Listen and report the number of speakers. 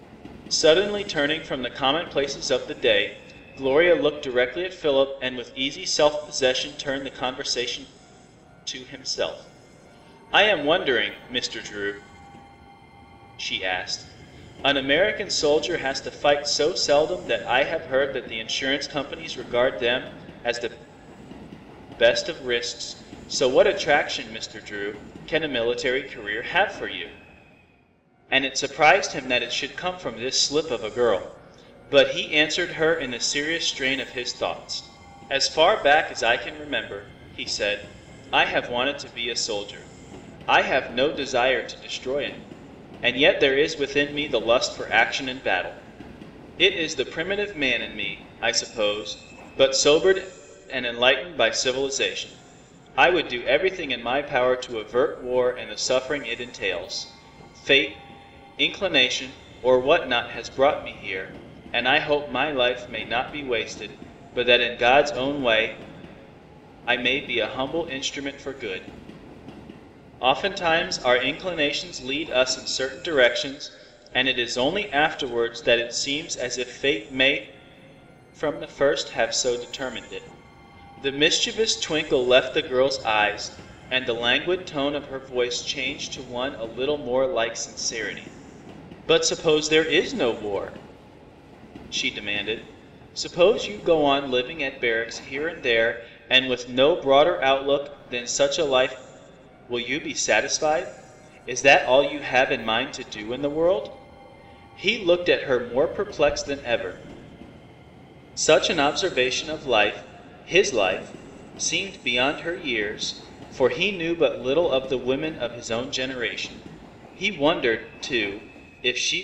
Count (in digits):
1